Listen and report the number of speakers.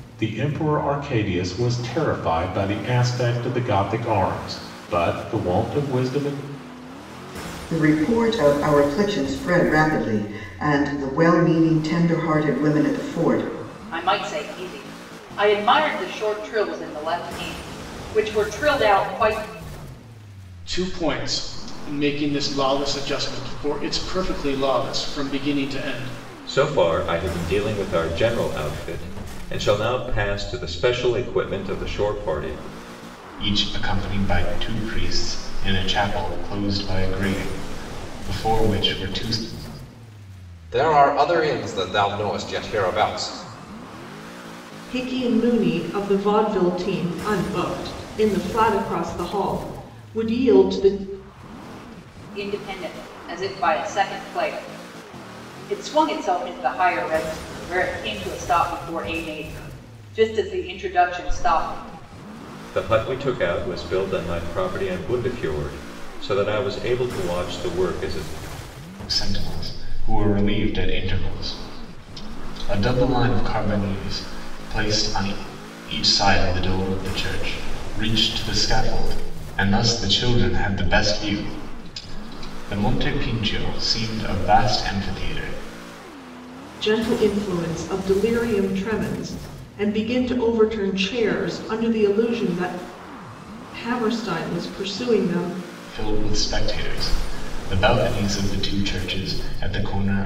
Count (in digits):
8